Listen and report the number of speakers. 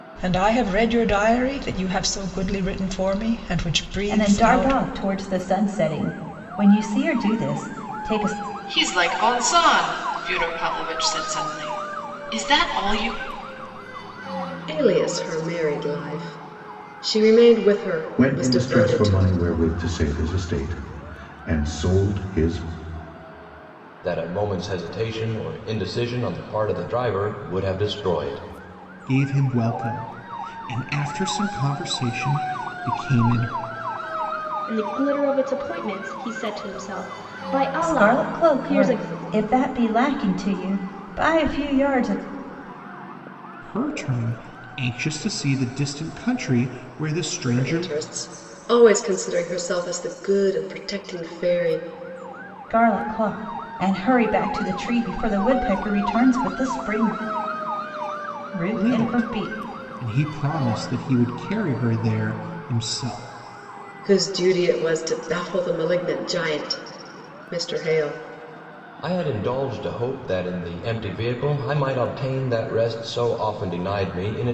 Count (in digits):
8